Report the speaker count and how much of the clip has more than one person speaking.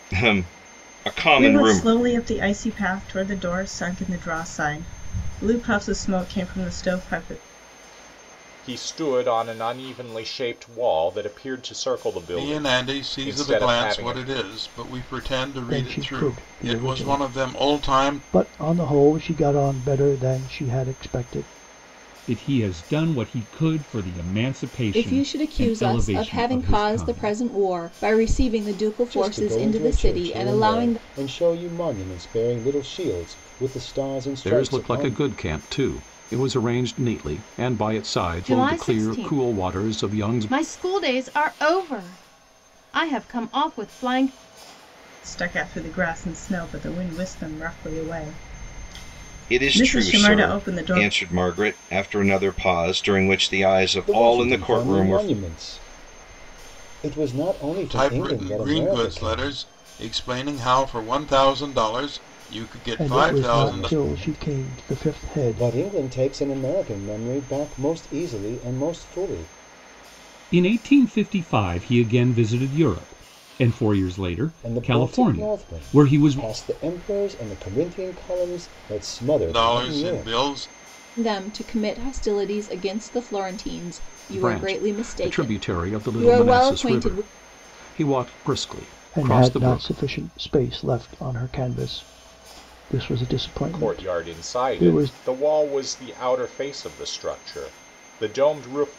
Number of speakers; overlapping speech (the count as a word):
ten, about 29%